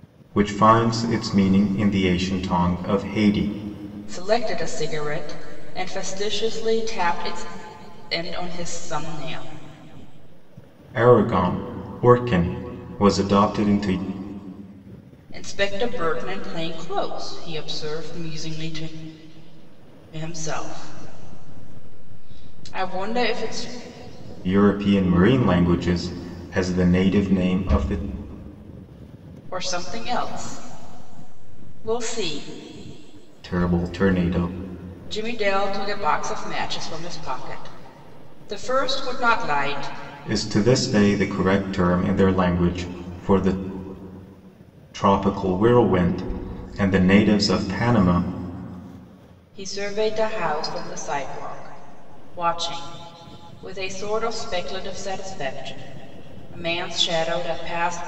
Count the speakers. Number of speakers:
2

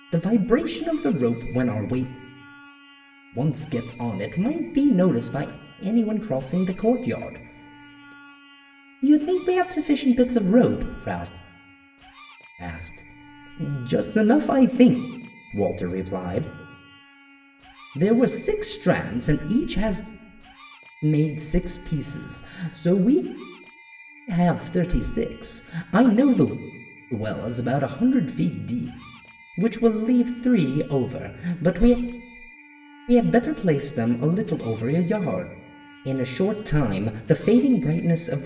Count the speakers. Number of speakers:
1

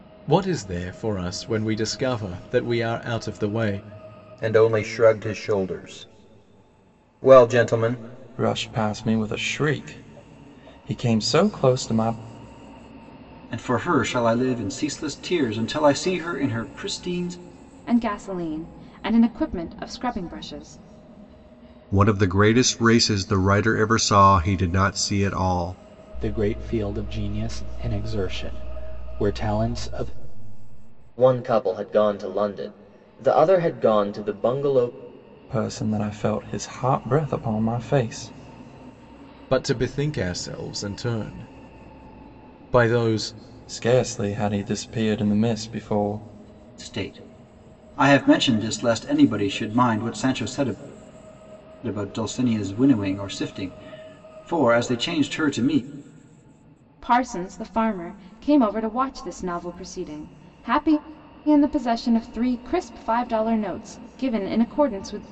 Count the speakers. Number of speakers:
8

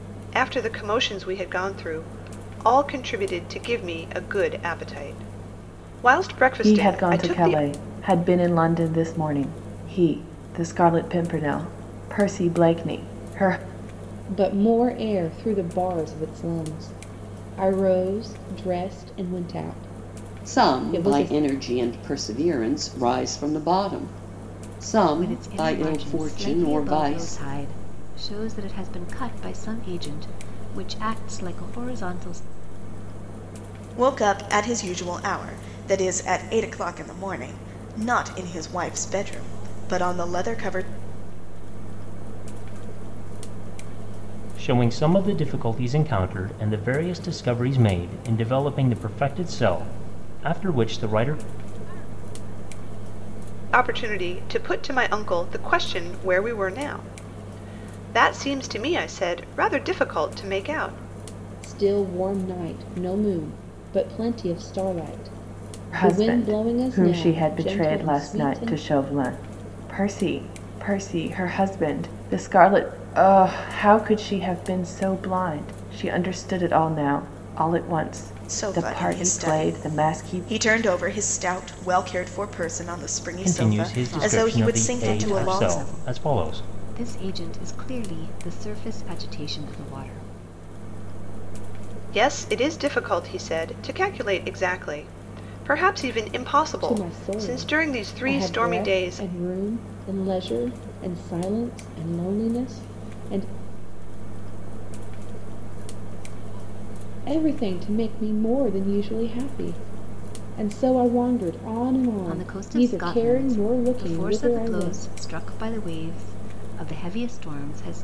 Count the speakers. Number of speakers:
8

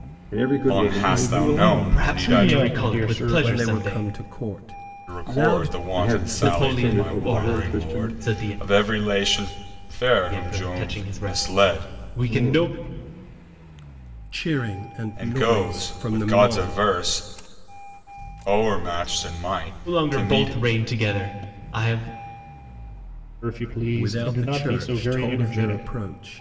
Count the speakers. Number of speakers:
5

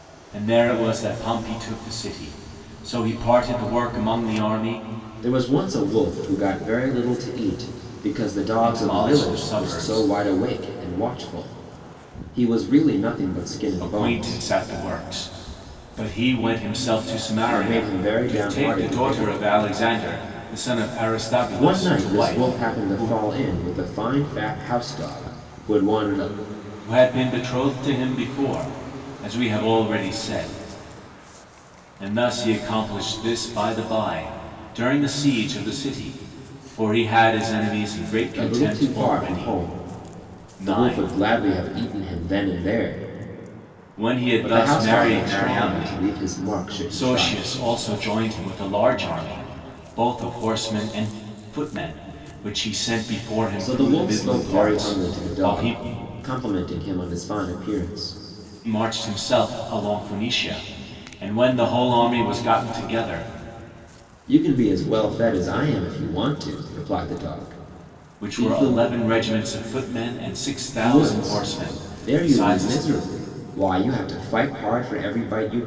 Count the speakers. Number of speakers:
2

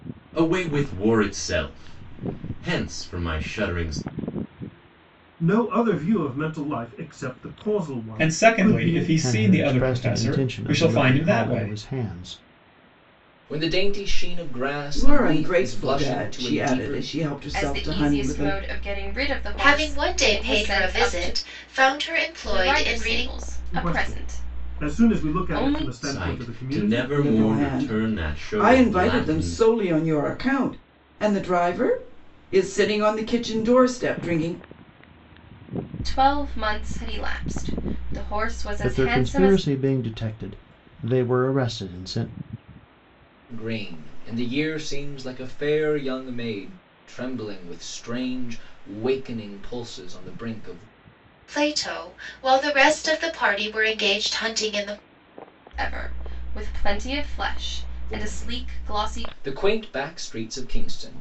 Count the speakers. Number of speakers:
8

